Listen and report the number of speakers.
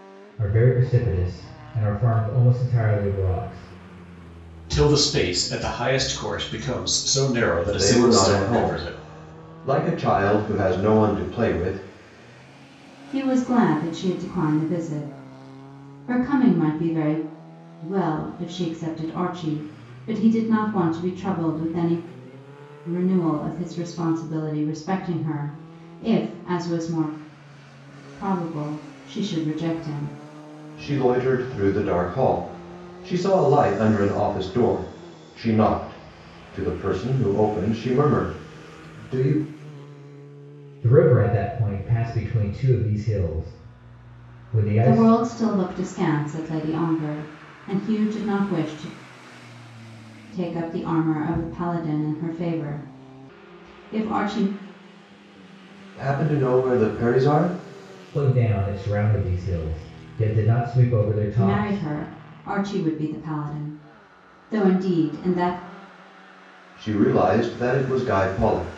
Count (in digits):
4